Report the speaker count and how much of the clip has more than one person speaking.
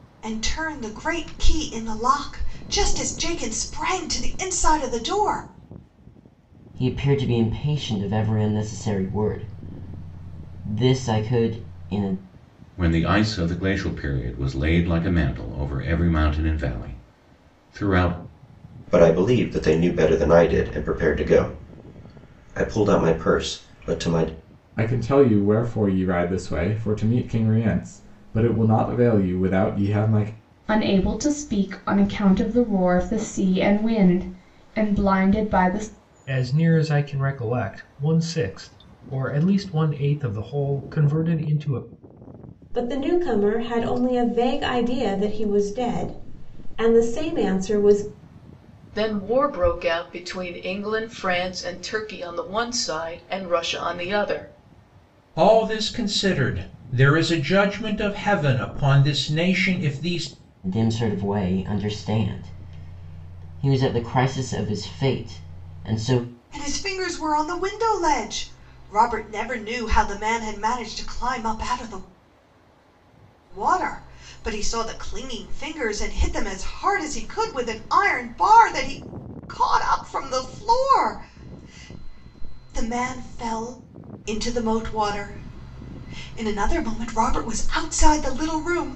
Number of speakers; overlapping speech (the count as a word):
ten, no overlap